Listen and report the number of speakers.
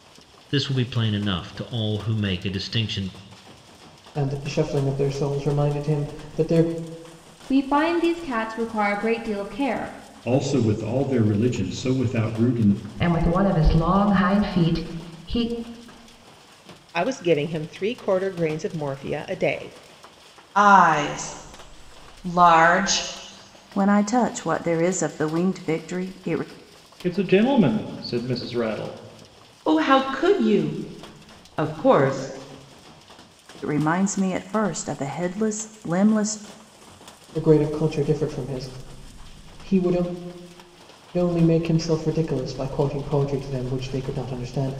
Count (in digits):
10